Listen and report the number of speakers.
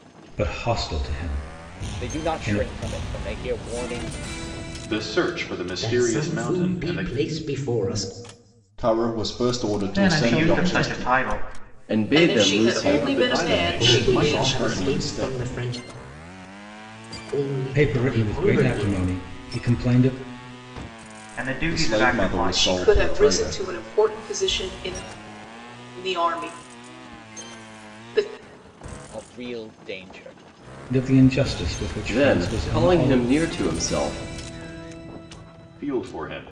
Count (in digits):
9